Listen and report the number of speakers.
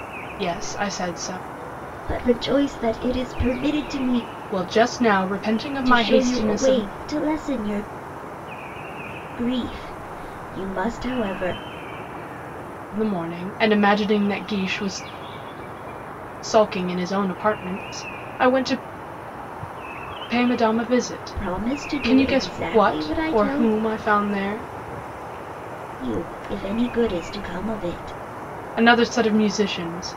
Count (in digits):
2